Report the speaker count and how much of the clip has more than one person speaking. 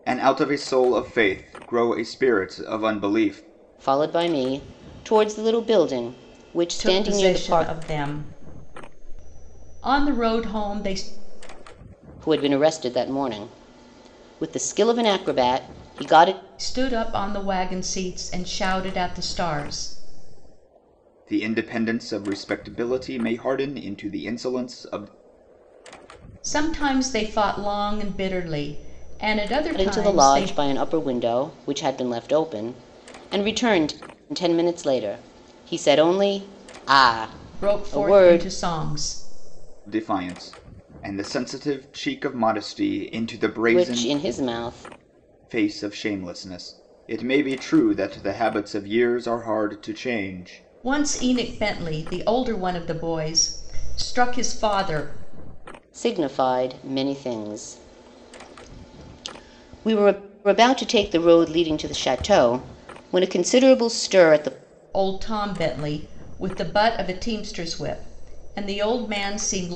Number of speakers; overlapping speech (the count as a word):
three, about 5%